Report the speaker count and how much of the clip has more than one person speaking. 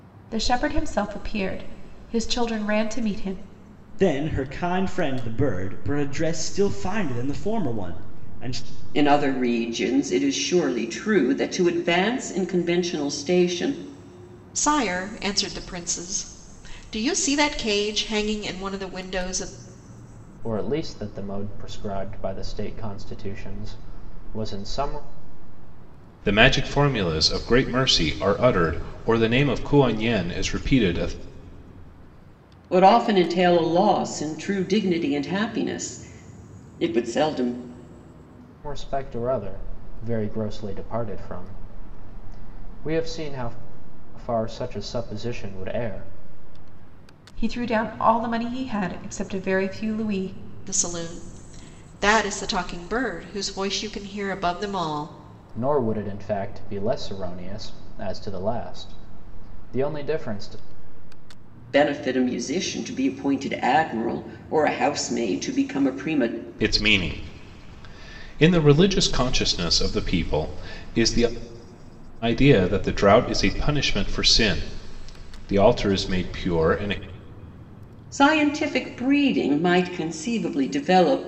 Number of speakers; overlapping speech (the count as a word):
six, no overlap